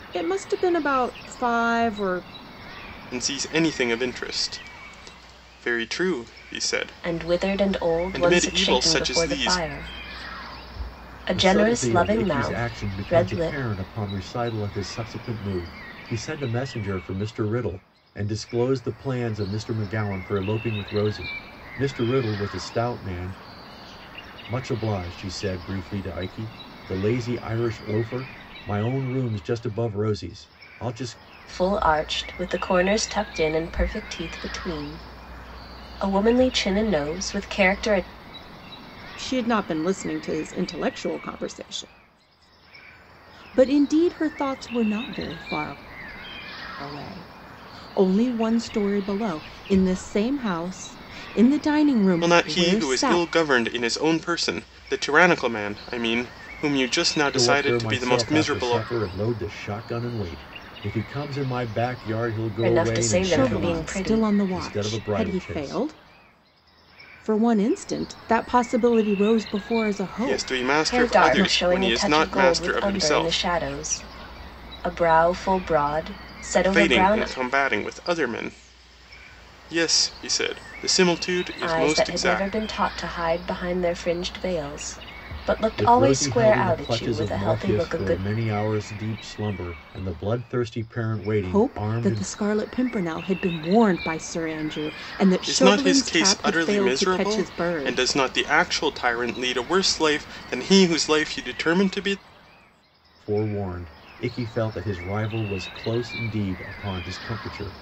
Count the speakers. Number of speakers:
four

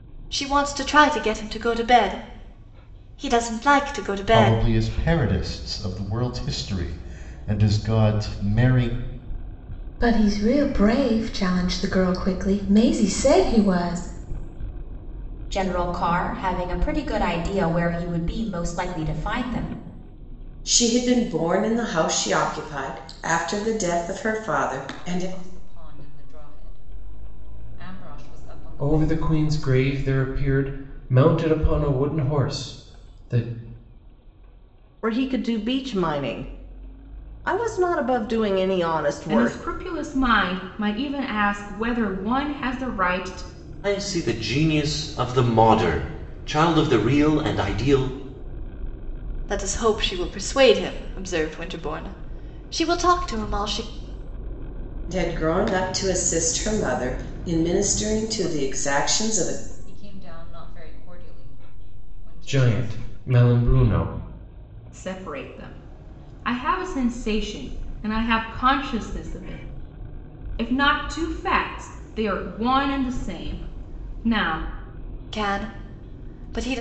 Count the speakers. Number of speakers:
ten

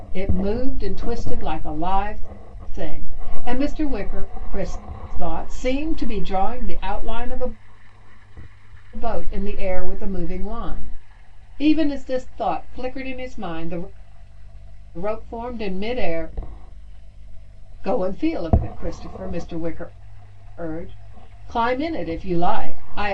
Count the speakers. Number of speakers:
one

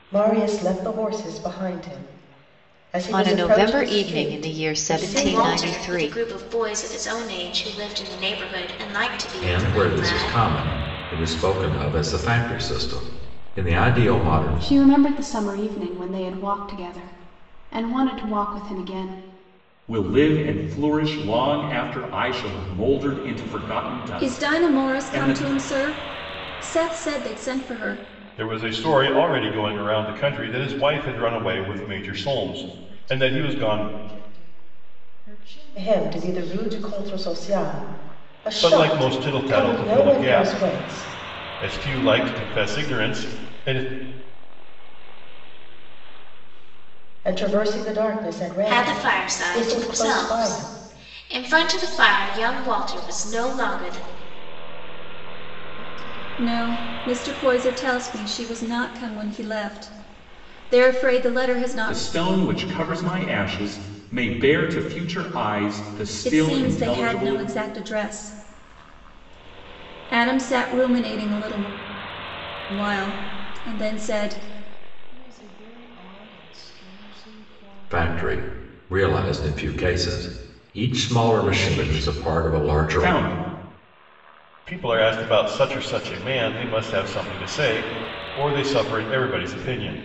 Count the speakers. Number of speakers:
ten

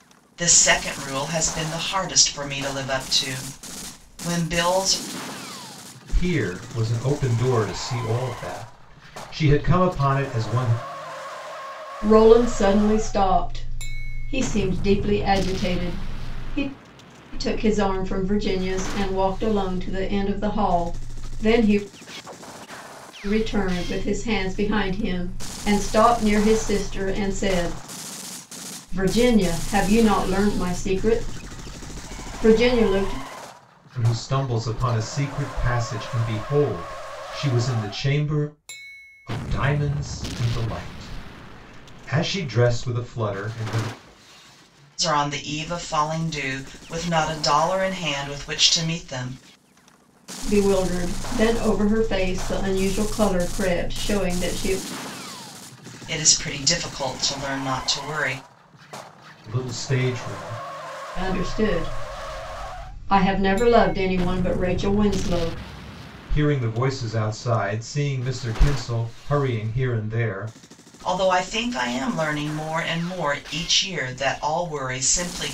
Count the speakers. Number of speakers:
three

